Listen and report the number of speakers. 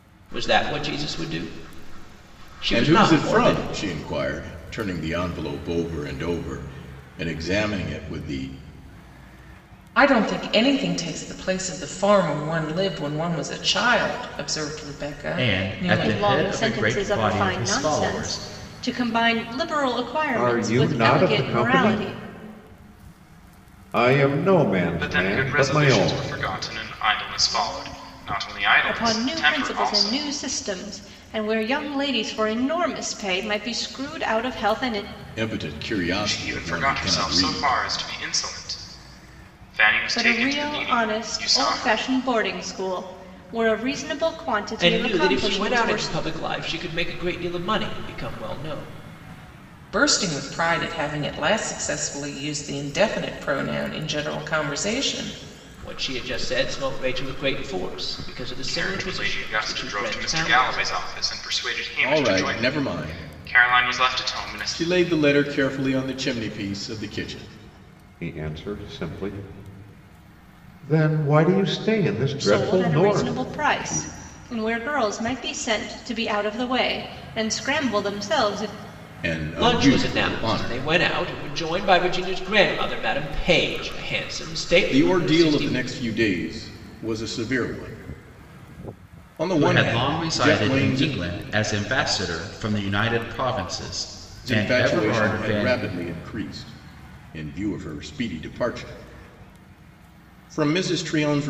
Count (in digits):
7